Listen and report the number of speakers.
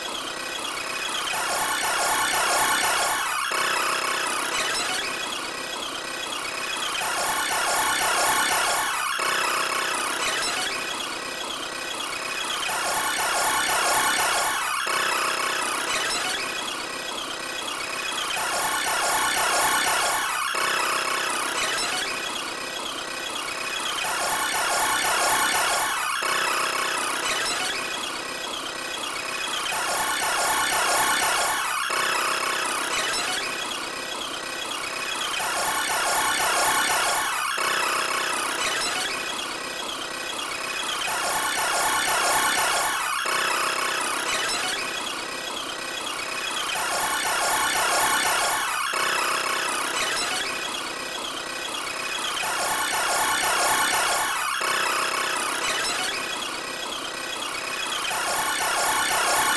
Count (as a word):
zero